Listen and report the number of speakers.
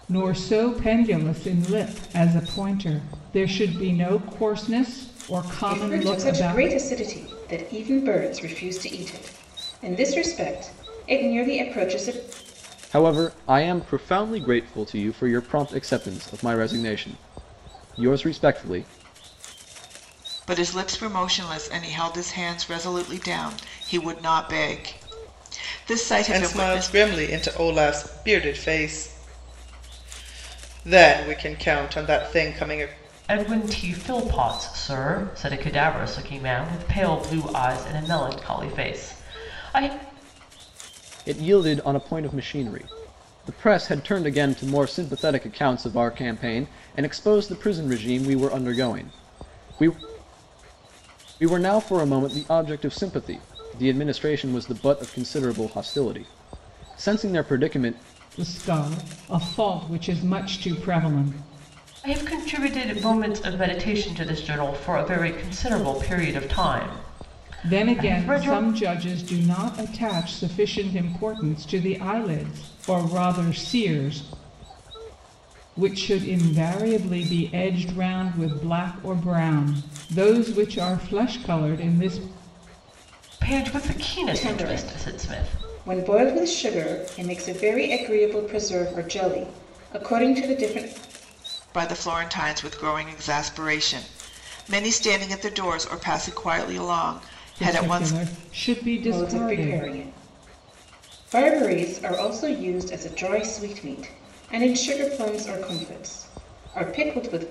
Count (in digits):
6